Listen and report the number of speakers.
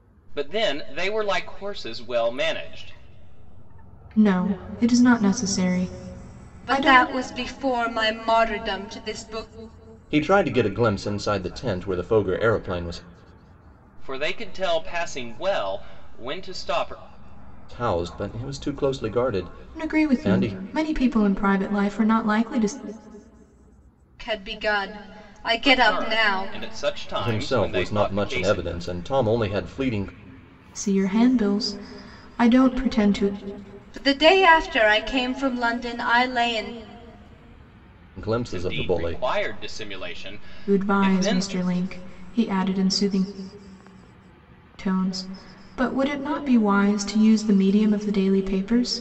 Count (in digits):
4